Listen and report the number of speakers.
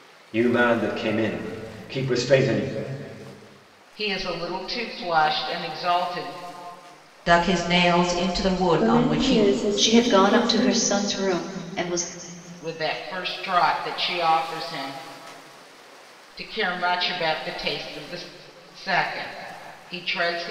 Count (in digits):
5